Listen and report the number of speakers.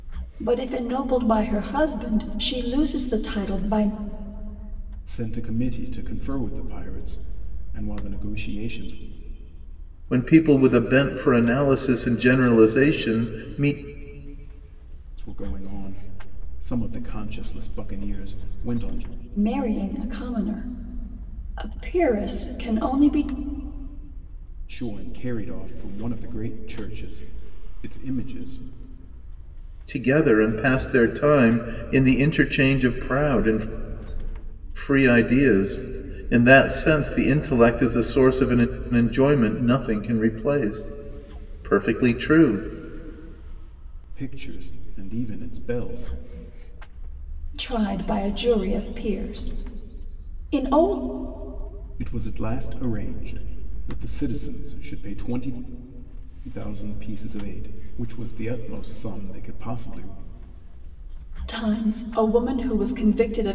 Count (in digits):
3